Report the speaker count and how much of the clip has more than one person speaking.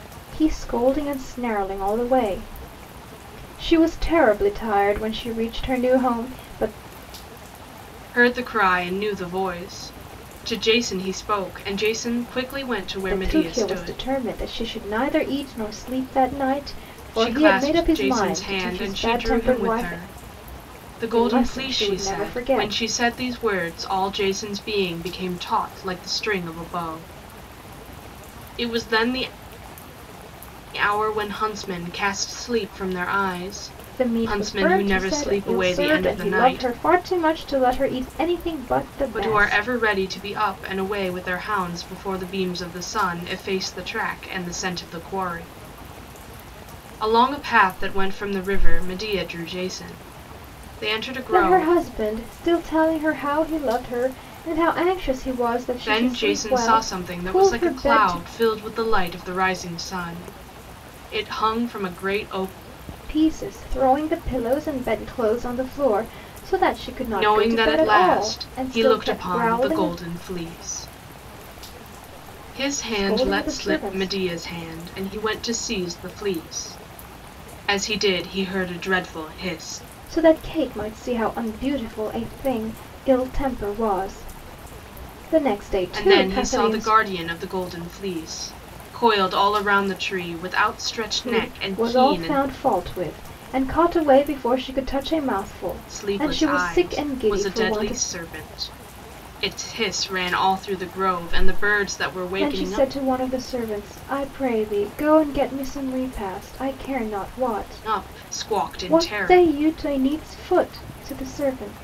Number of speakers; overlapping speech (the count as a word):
two, about 21%